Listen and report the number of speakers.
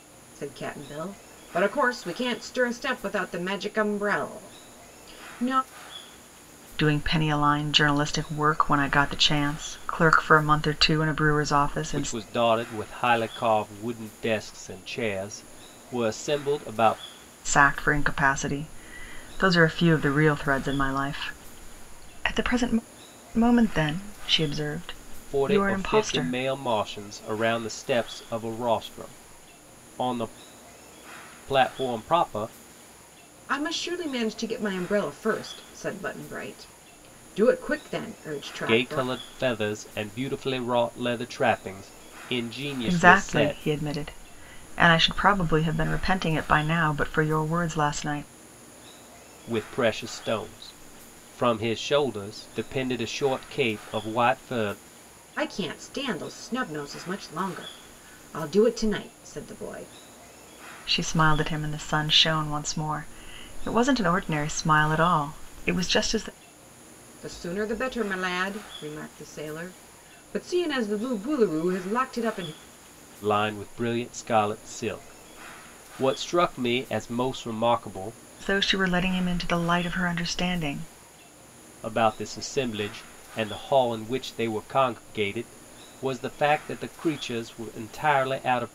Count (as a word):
three